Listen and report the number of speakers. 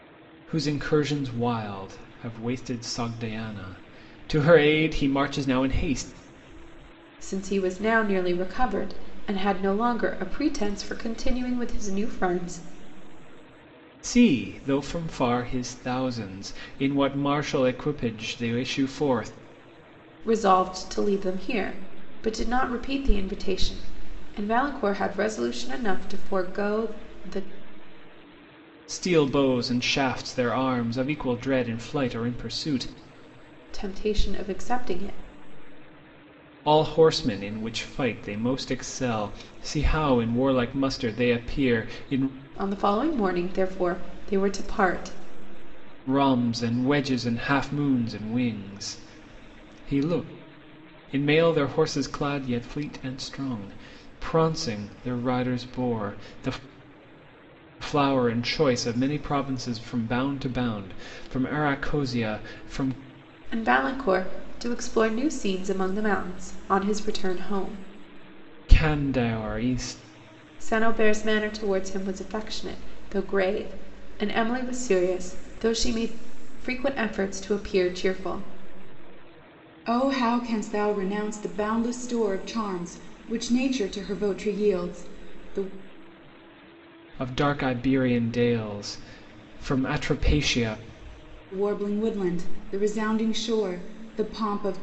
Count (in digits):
2